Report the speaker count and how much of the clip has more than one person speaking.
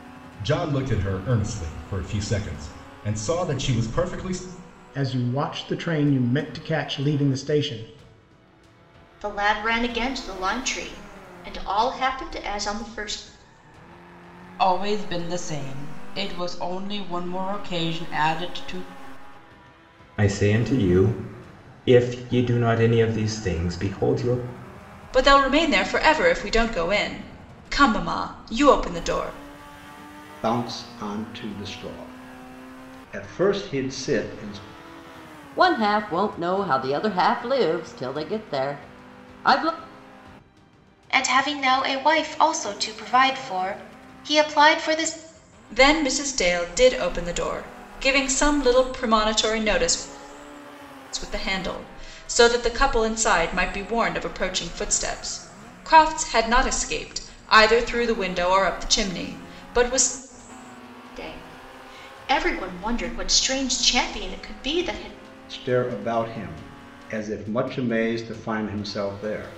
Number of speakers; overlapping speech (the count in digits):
9, no overlap